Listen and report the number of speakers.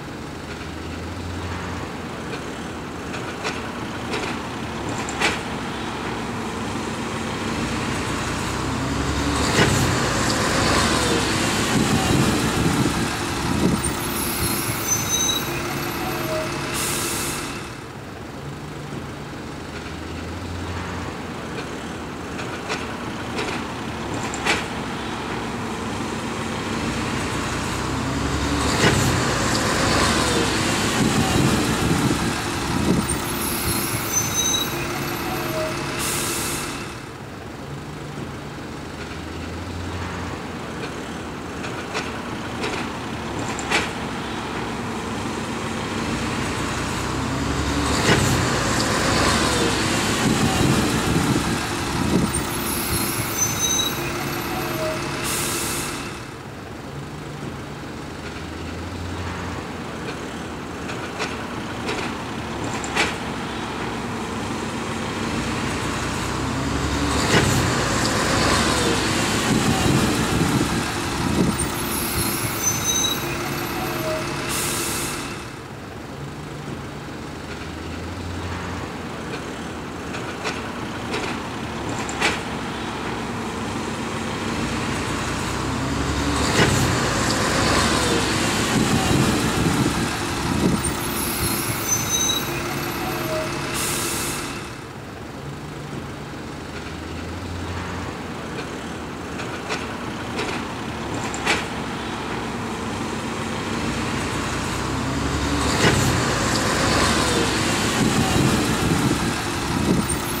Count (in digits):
0